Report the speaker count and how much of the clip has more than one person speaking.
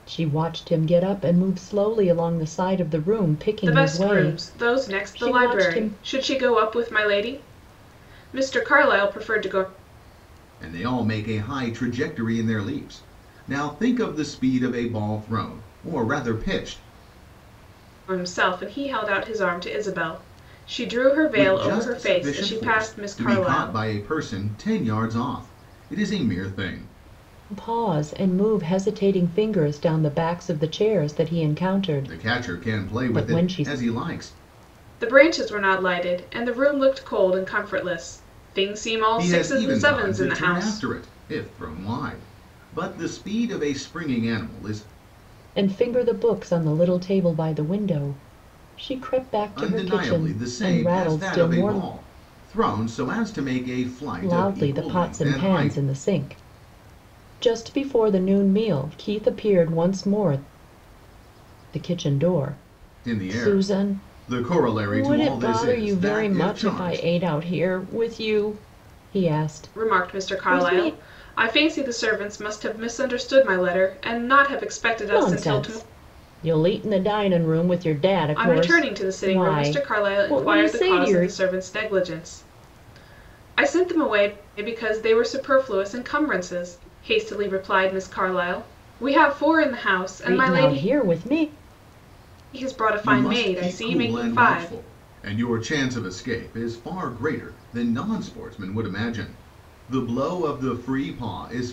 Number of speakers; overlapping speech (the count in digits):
3, about 22%